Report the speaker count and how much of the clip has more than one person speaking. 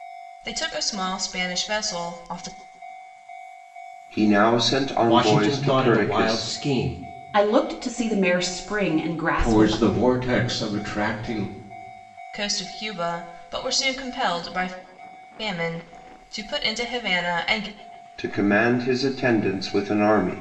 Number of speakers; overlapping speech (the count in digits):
5, about 9%